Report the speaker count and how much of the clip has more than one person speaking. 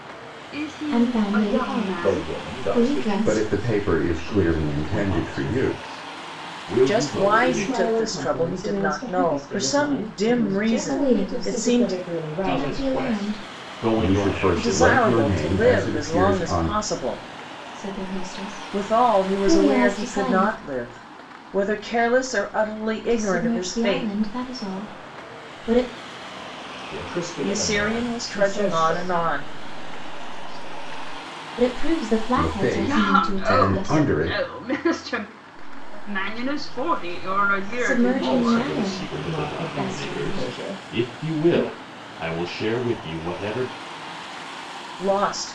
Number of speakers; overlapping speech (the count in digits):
8, about 60%